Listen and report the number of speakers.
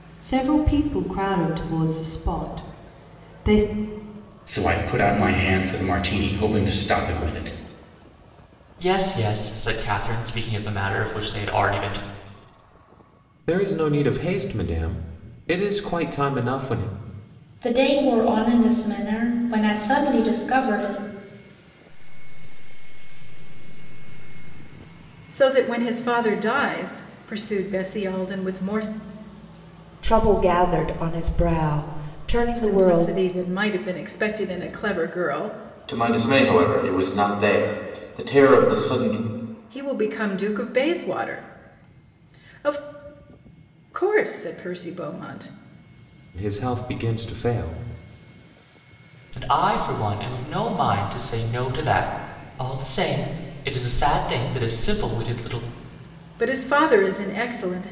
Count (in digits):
8